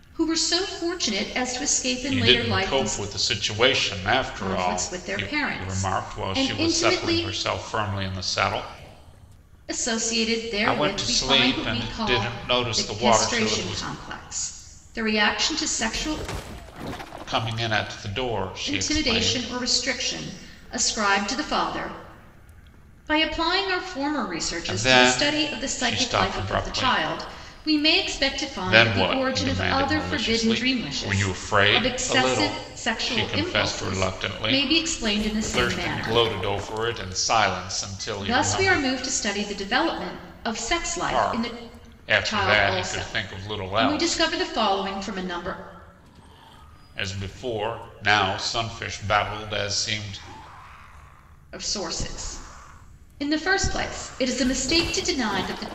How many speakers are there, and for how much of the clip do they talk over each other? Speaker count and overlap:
2, about 36%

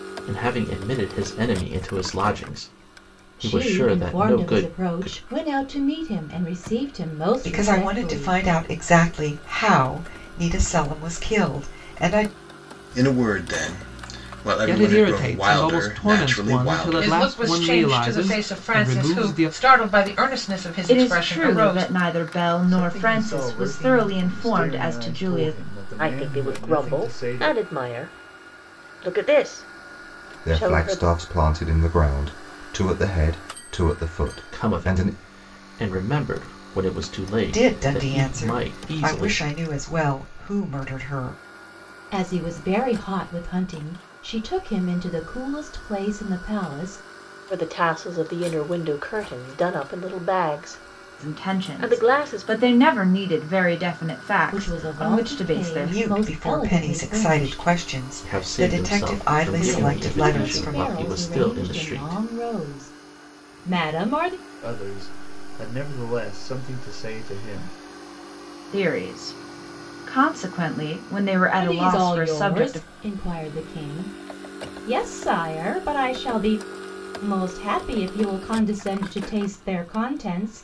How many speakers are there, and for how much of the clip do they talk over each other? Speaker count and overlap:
10, about 33%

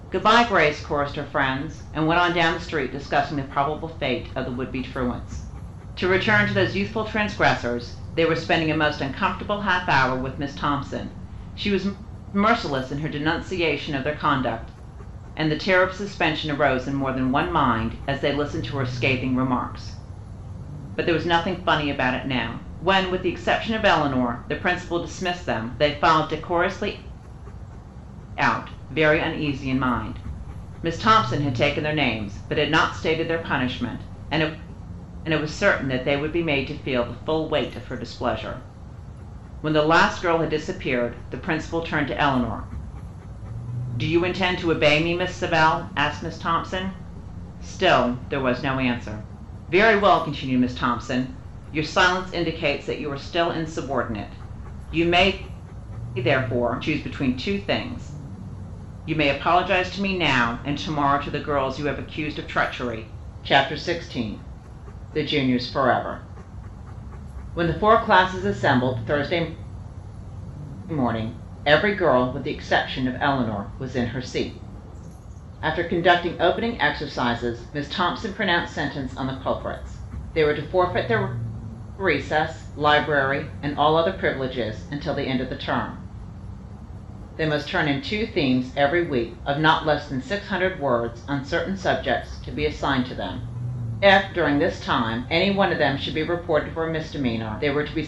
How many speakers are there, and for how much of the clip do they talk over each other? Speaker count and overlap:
1, no overlap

